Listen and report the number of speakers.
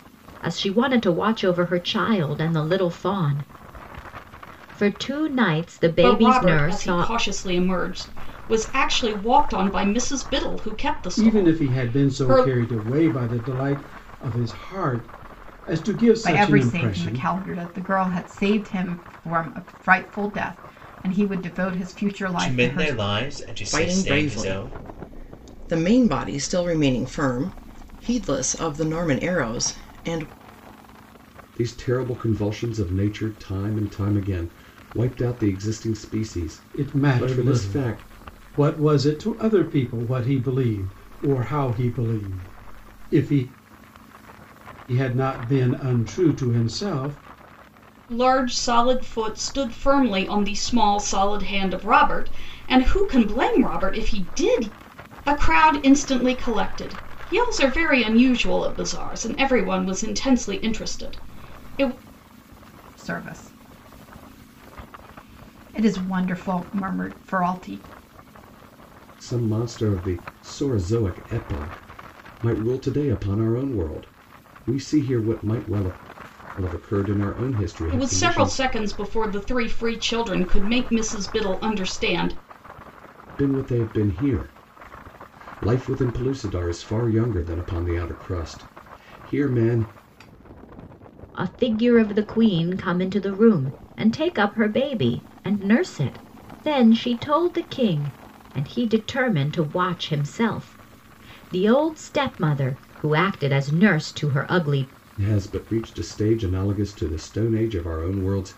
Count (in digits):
7